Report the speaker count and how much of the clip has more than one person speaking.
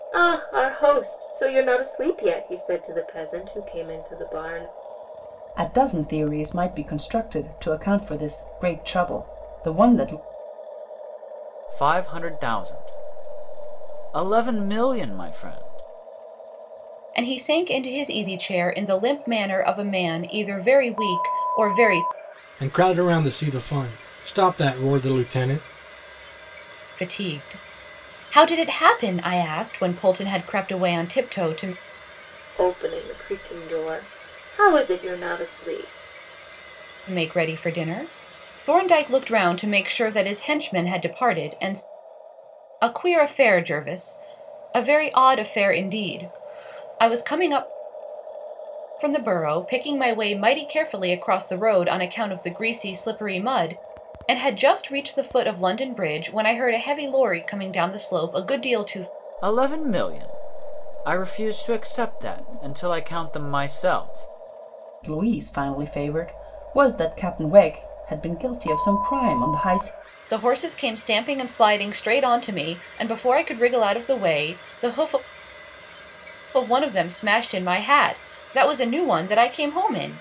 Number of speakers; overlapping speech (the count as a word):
five, no overlap